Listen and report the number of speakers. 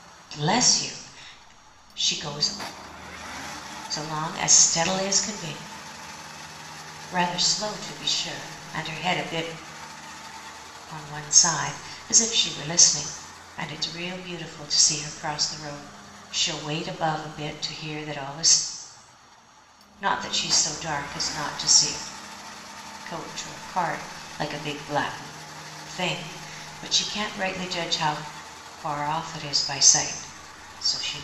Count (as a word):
one